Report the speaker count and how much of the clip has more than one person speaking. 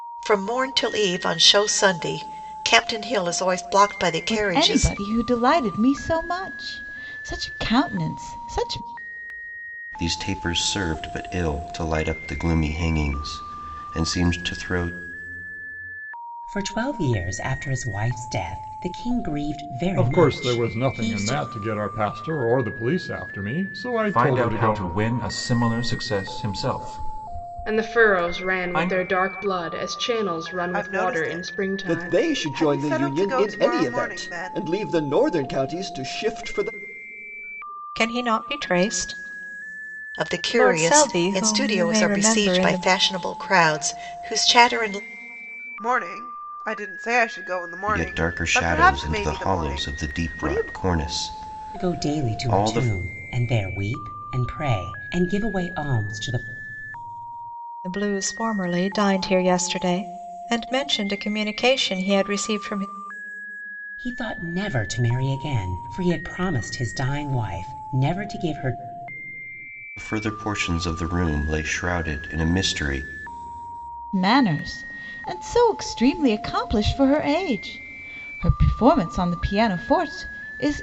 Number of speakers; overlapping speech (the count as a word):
ten, about 18%